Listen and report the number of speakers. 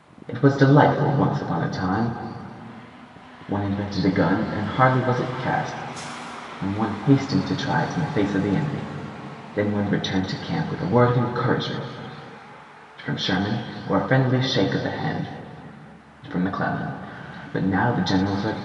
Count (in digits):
1